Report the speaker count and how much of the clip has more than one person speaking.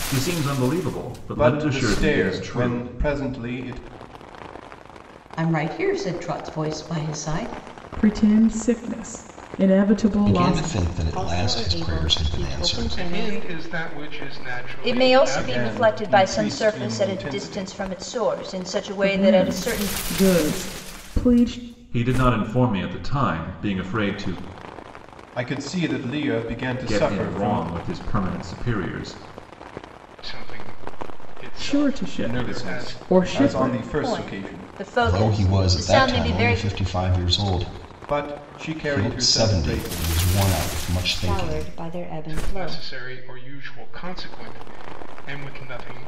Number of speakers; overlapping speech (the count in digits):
8, about 35%